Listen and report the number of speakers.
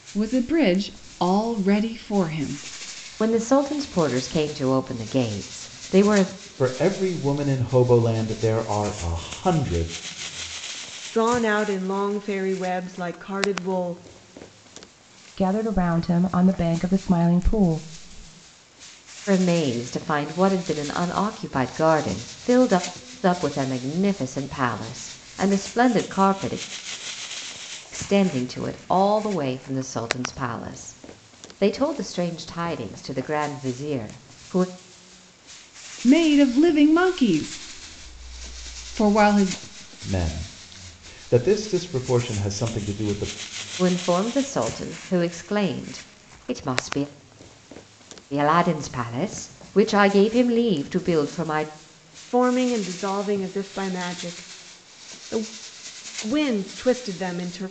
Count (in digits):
5